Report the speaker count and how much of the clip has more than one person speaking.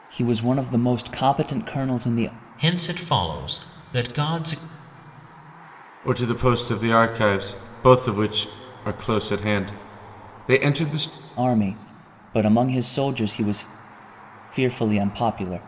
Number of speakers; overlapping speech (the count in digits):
3, no overlap